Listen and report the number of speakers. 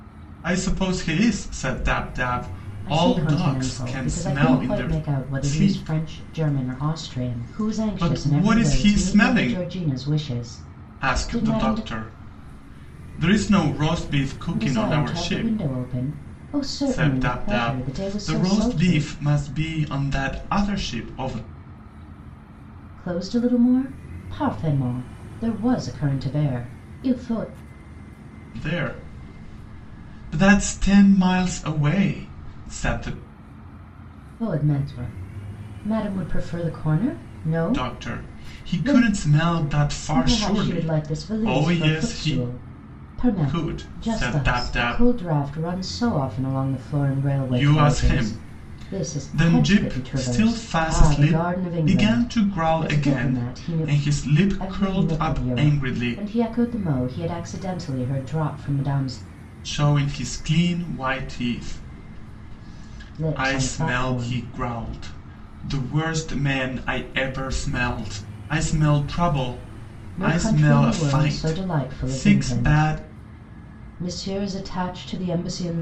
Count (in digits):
2